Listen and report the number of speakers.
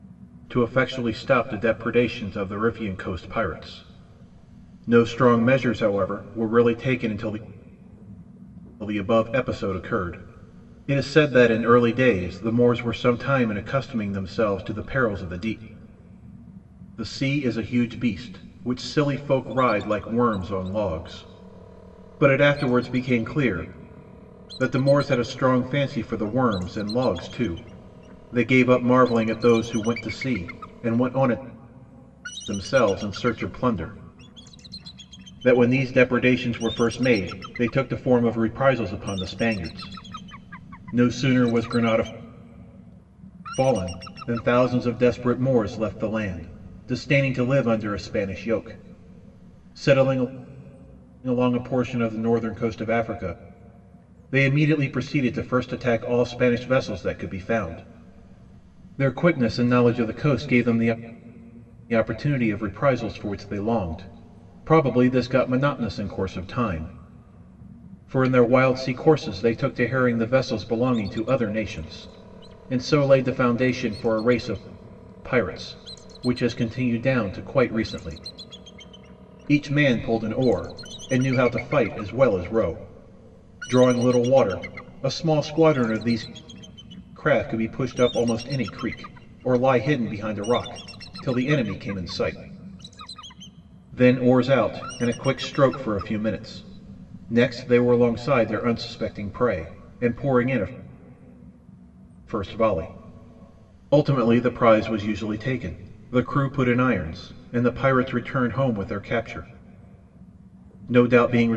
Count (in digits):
1